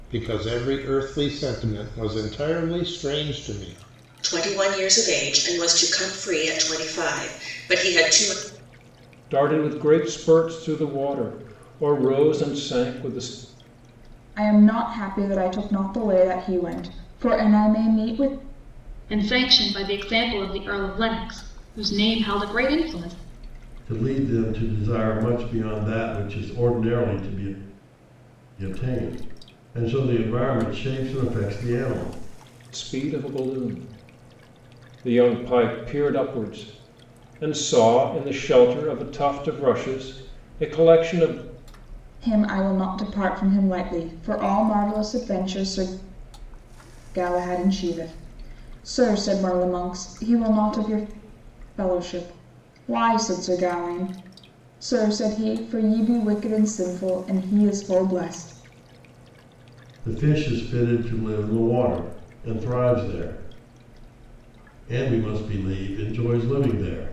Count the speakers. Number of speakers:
6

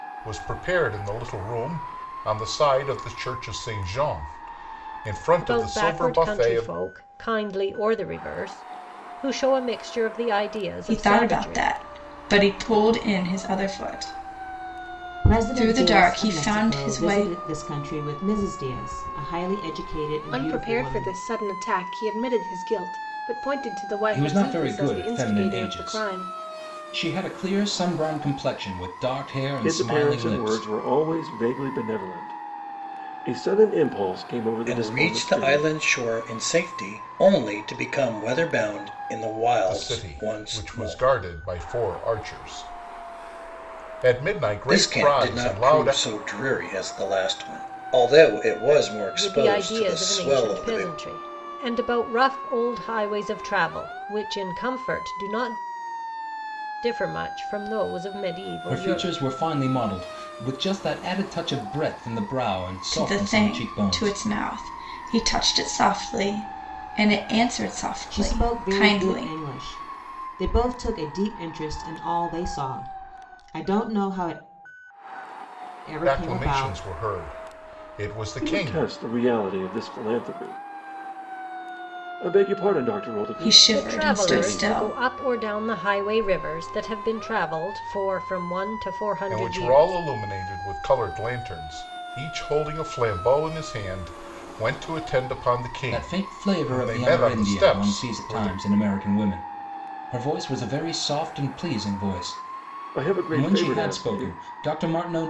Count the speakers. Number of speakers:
8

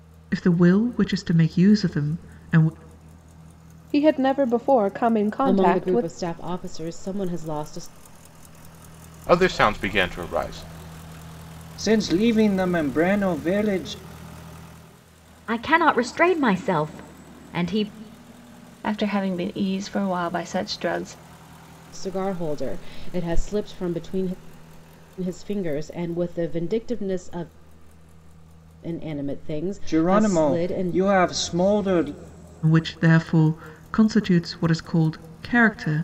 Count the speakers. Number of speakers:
7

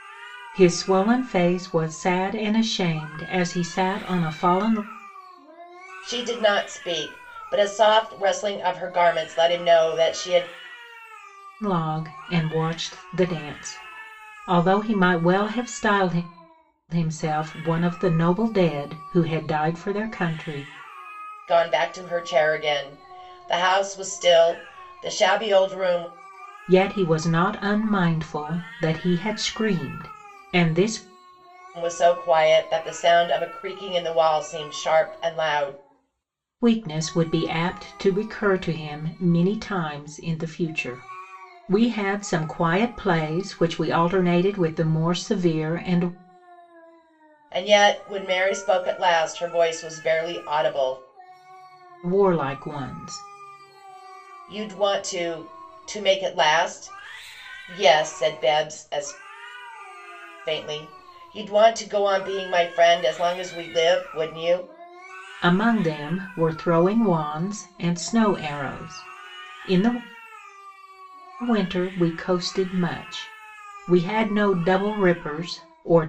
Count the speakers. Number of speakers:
2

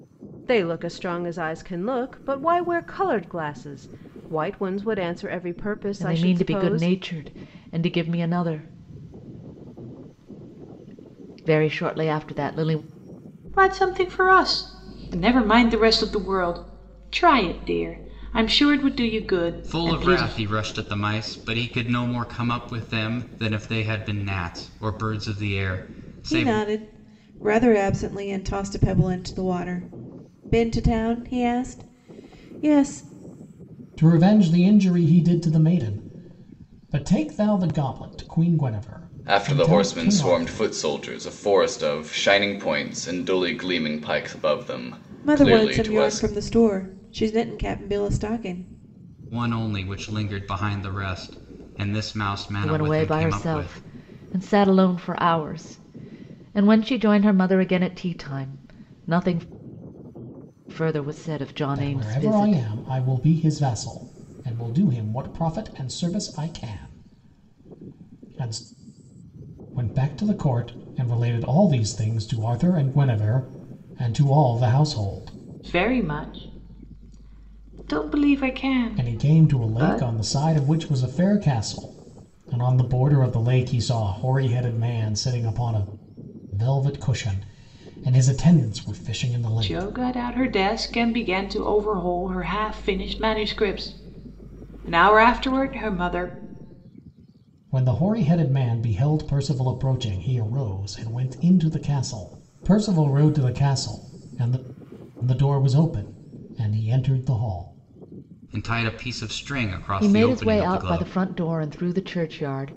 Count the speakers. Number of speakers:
7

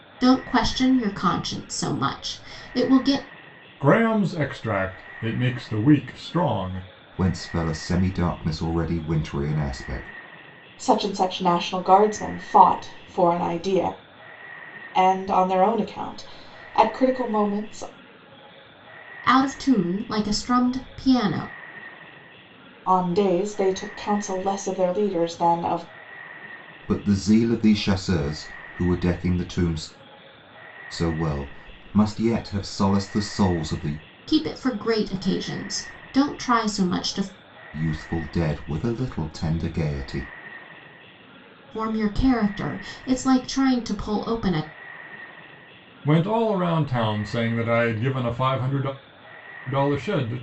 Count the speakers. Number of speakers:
4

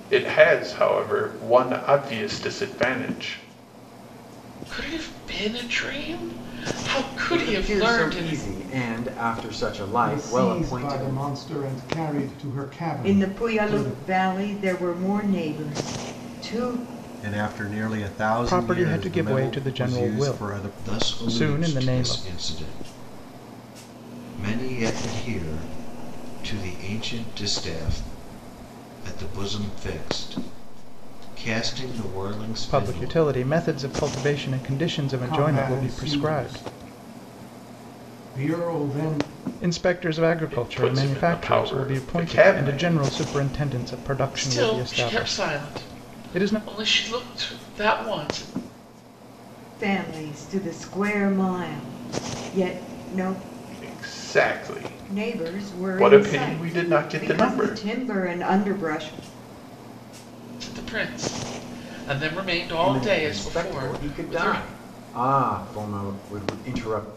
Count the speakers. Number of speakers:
8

